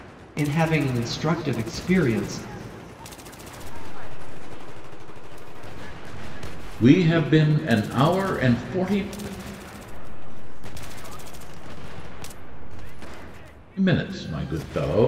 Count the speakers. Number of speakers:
3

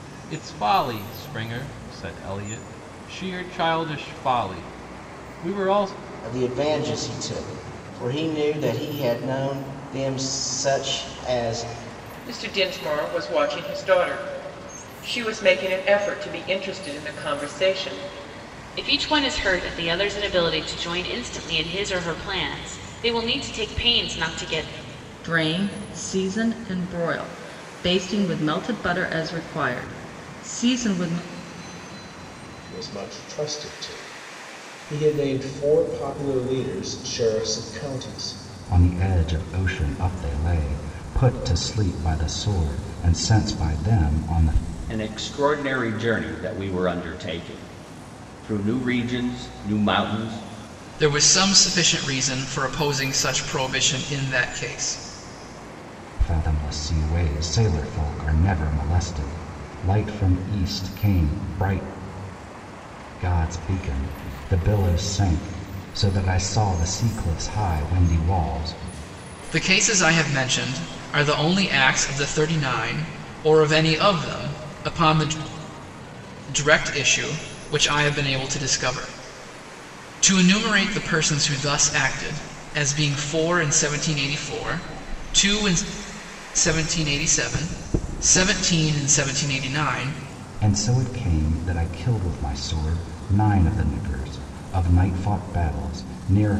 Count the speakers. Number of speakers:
9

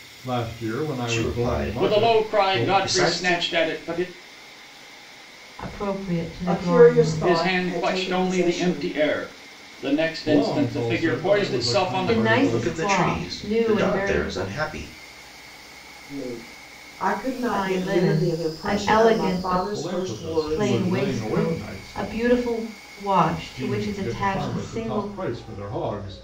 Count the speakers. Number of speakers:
5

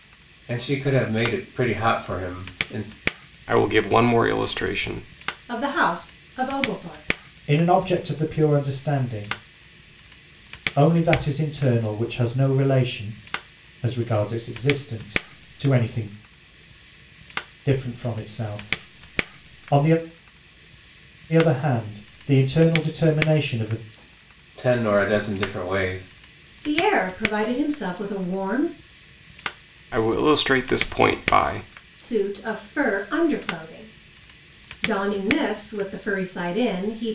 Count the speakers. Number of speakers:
4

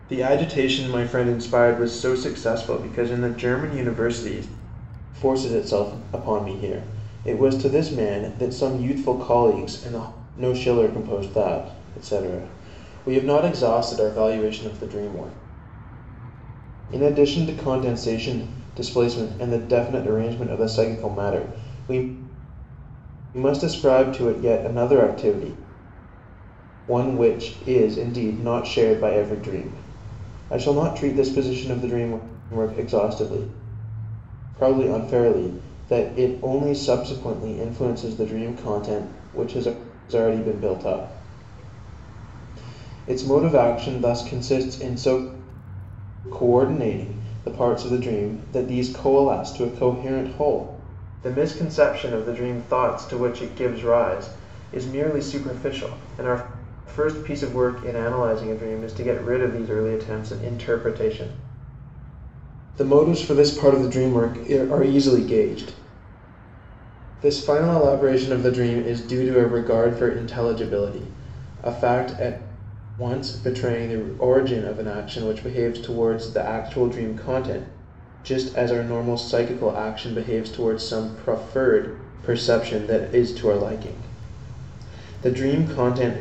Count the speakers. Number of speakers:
1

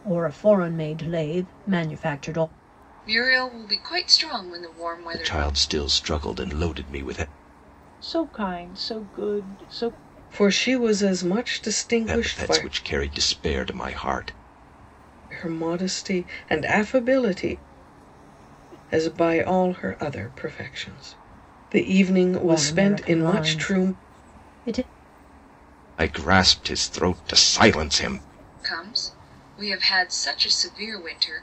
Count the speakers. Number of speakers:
5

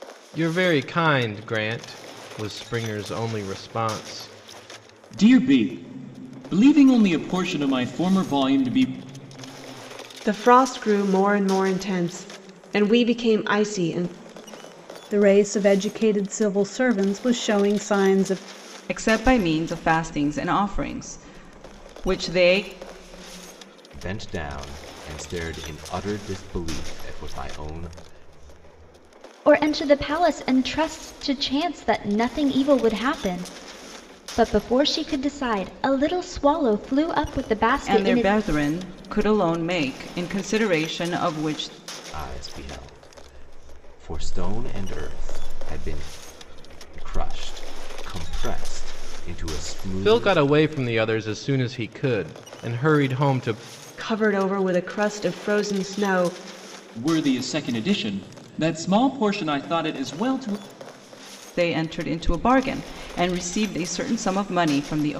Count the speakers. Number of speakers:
7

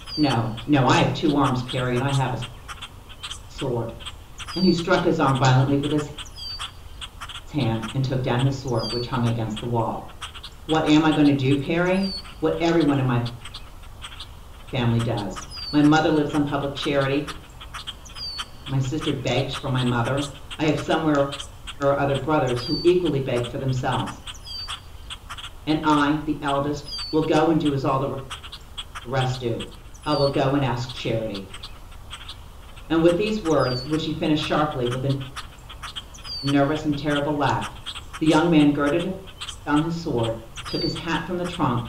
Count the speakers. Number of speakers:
1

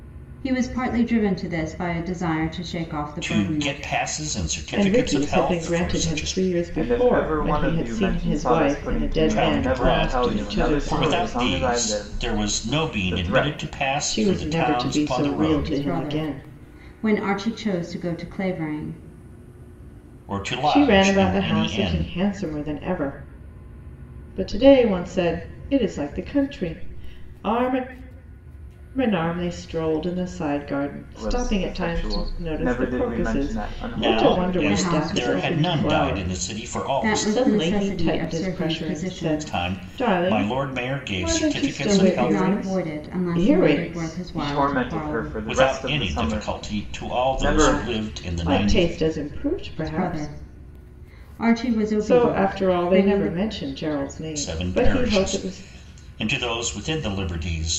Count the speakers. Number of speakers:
4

